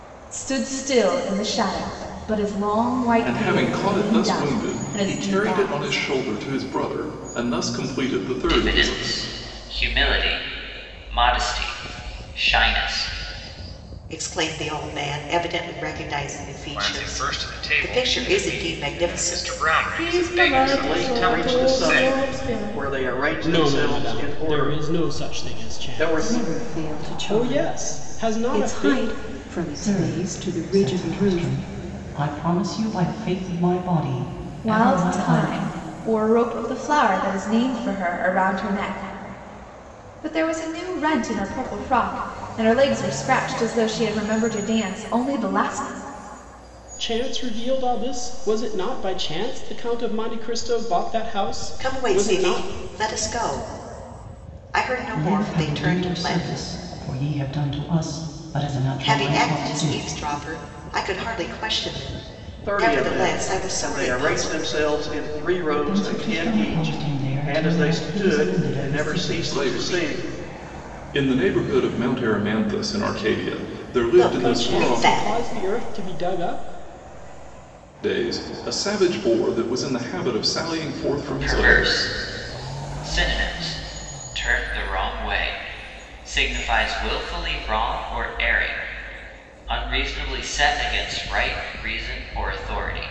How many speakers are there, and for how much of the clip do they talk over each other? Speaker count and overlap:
10, about 32%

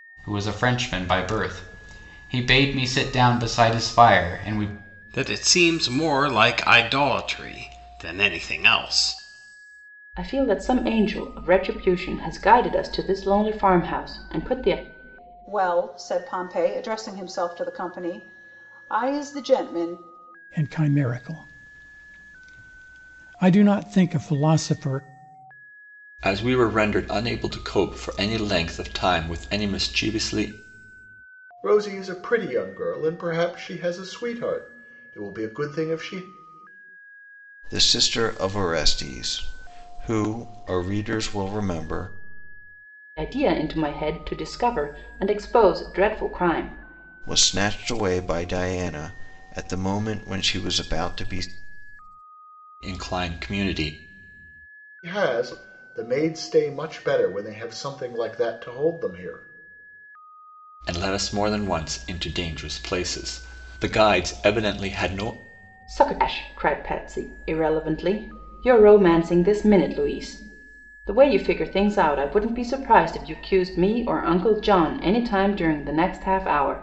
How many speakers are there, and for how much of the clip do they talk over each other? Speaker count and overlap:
8, no overlap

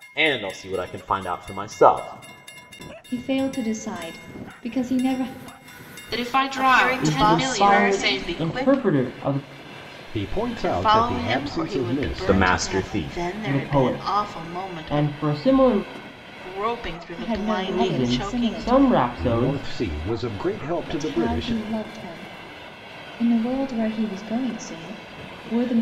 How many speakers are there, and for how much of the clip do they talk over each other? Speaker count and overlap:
6, about 38%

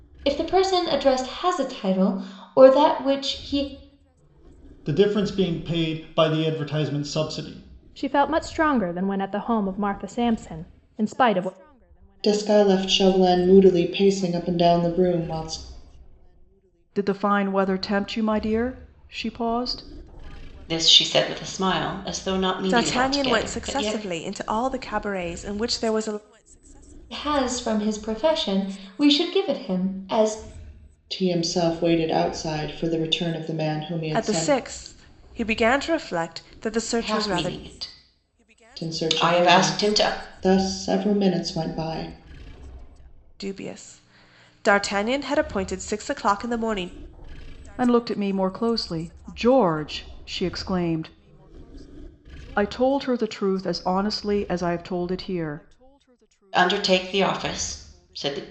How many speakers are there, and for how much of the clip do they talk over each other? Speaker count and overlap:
7, about 7%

